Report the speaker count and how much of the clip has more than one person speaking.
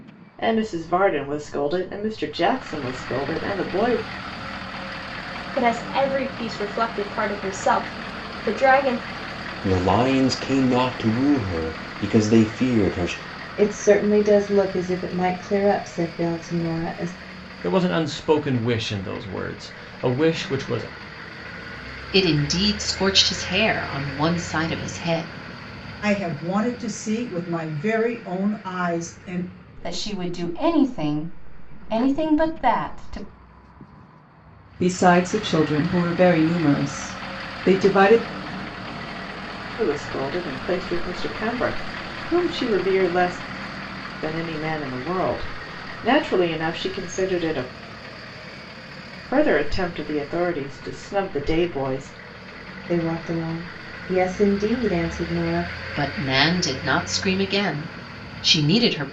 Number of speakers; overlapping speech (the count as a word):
nine, no overlap